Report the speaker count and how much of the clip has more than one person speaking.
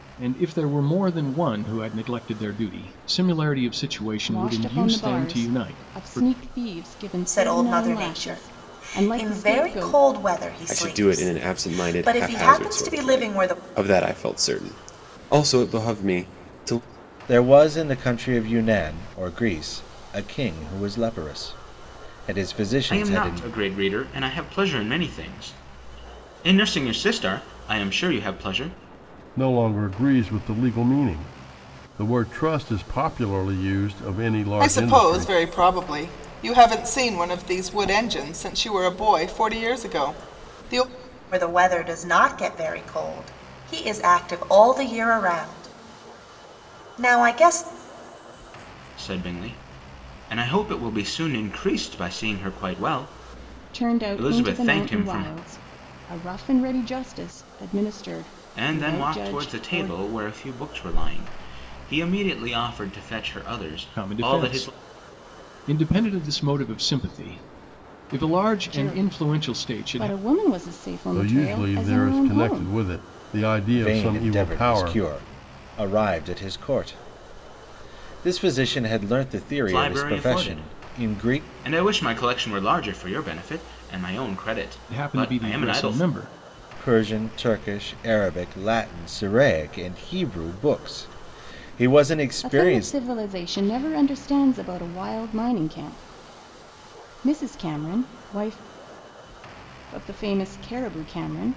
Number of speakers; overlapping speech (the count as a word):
eight, about 21%